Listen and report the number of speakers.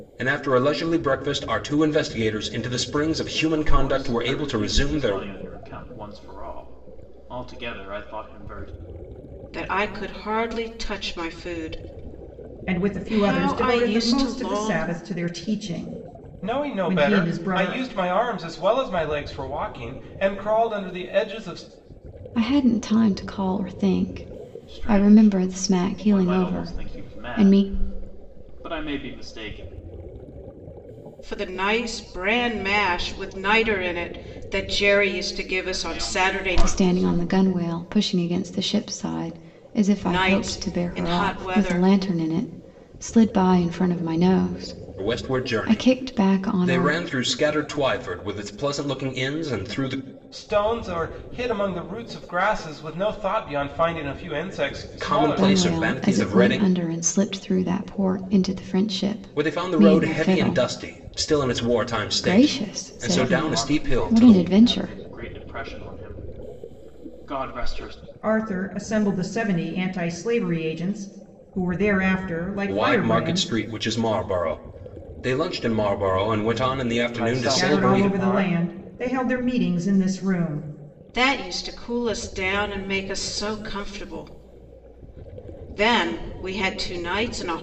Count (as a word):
six